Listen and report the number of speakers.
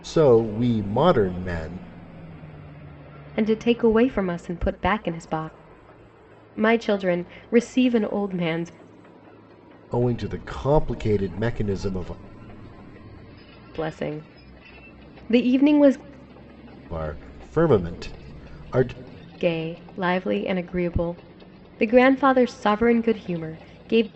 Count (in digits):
2